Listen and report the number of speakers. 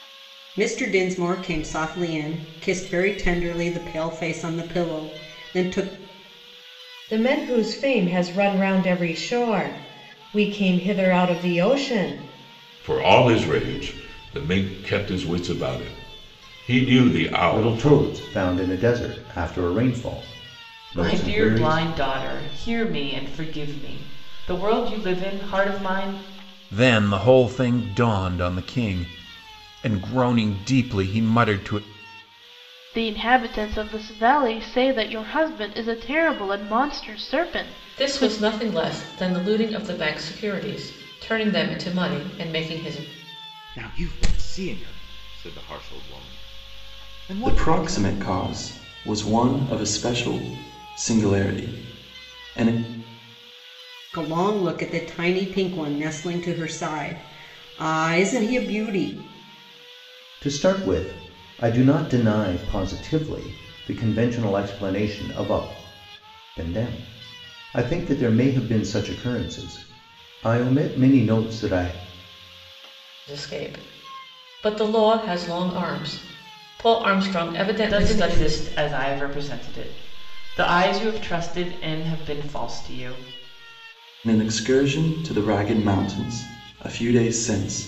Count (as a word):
ten